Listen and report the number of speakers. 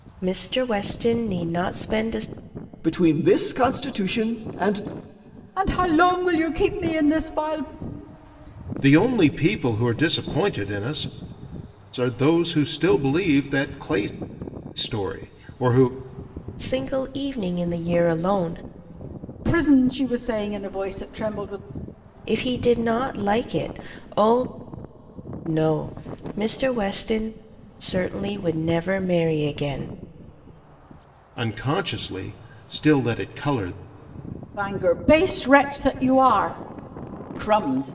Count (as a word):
four